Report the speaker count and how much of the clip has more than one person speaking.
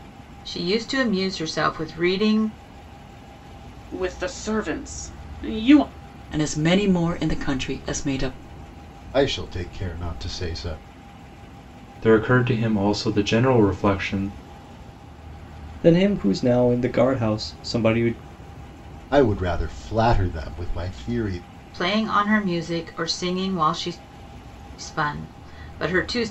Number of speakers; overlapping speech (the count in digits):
6, no overlap